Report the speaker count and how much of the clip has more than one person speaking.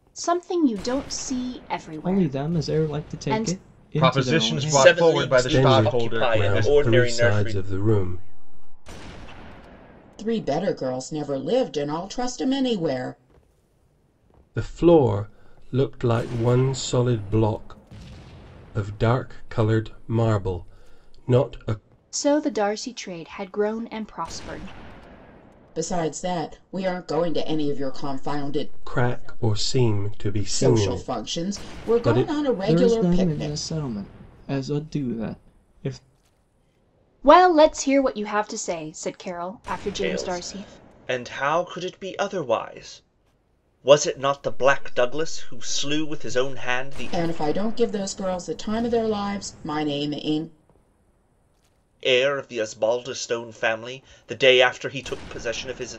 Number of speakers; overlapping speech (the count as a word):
seven, about 29%